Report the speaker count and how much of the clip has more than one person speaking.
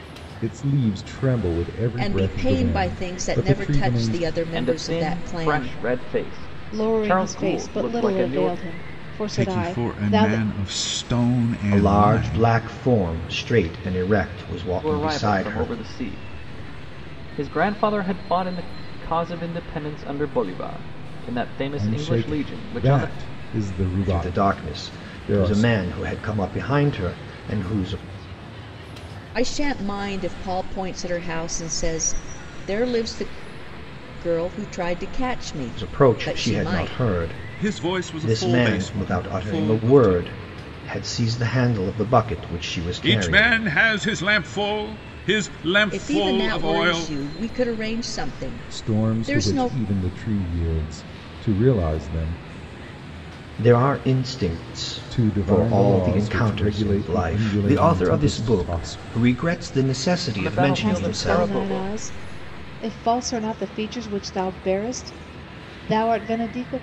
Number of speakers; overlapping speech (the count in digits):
6, about 36%